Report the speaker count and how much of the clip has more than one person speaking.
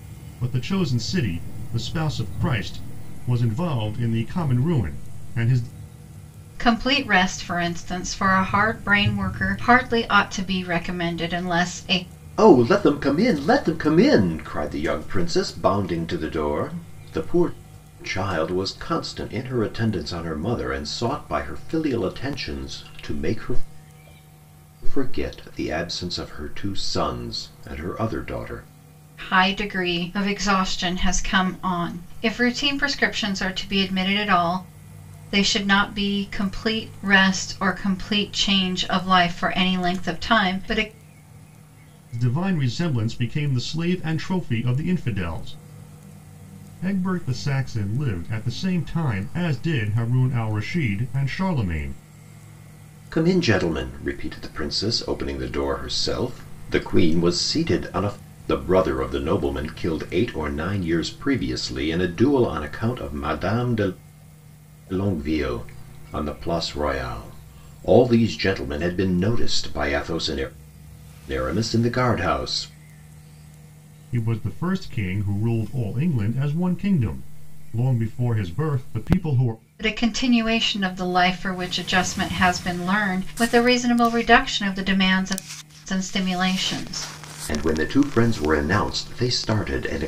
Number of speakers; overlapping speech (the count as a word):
three, no overlap